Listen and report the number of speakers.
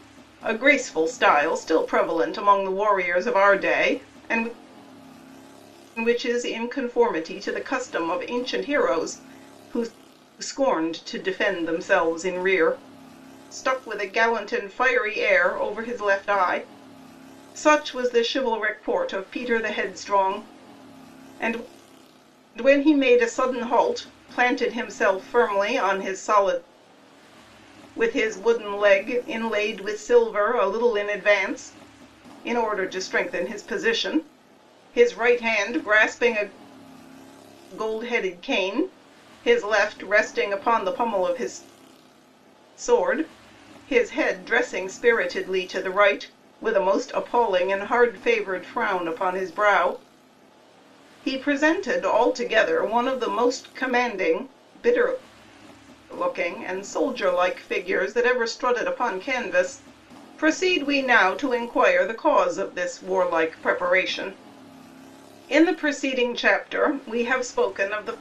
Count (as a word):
one